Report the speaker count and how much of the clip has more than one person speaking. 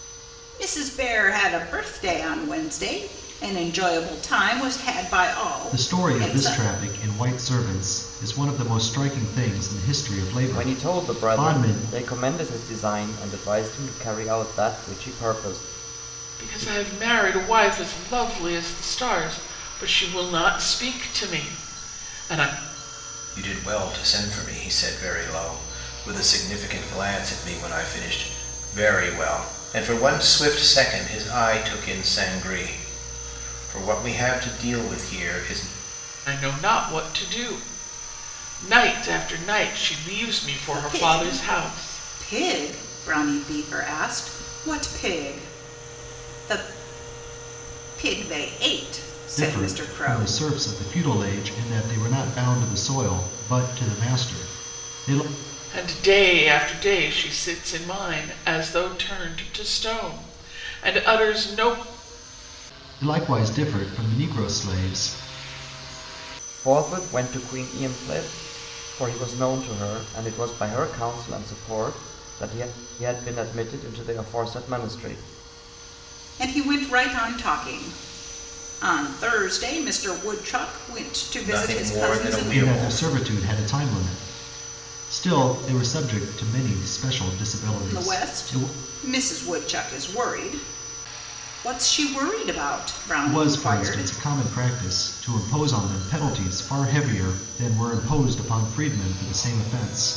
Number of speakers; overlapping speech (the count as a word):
five, about 9%